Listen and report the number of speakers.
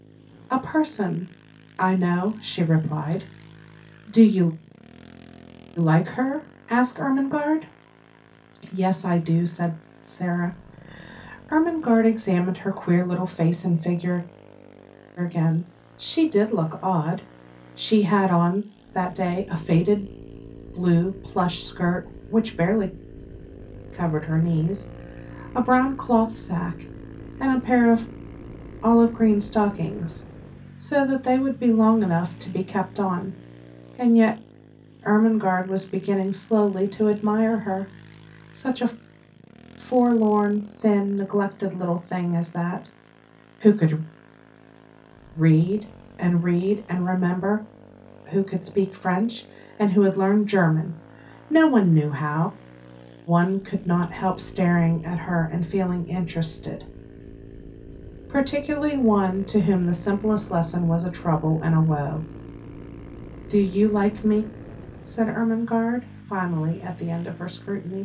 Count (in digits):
1